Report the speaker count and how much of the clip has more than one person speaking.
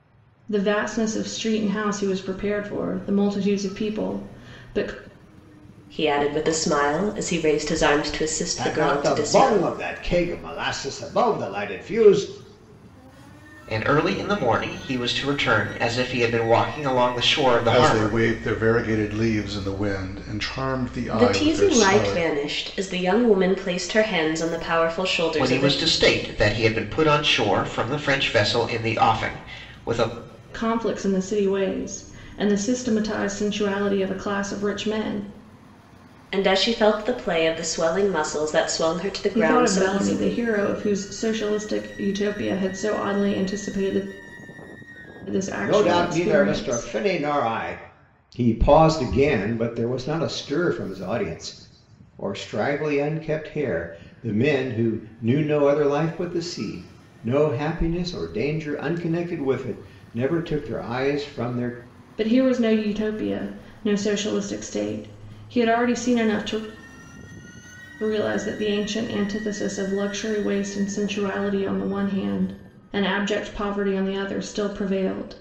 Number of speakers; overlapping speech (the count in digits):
5, about 8%